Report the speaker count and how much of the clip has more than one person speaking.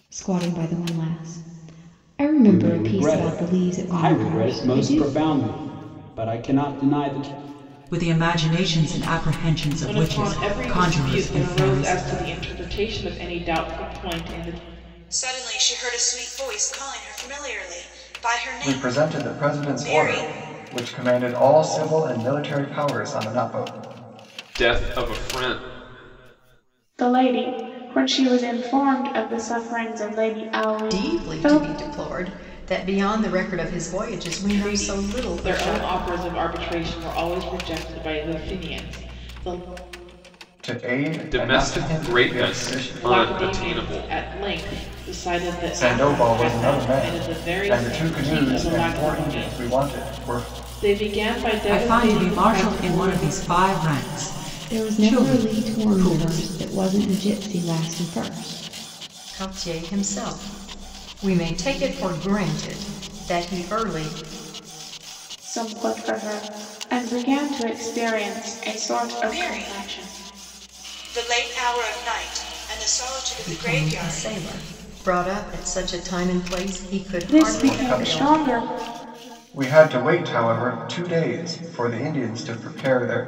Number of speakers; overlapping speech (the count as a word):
nine, about 28%